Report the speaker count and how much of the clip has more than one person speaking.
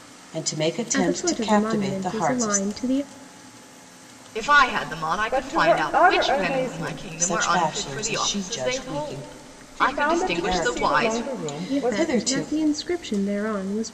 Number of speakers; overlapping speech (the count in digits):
4, about 61%